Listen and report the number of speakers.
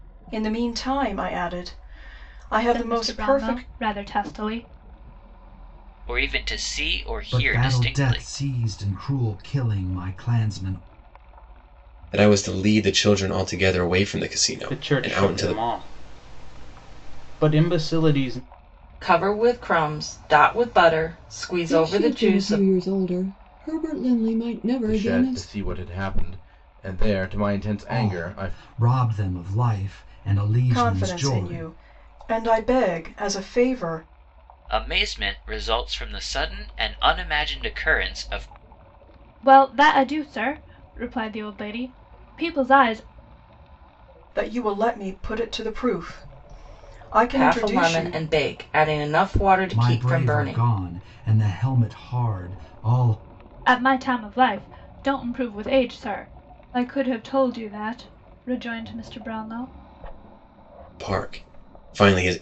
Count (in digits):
9